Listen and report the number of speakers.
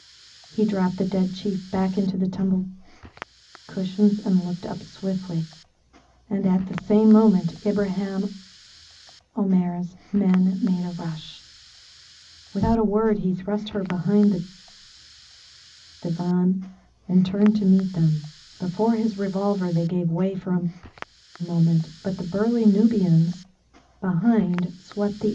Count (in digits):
1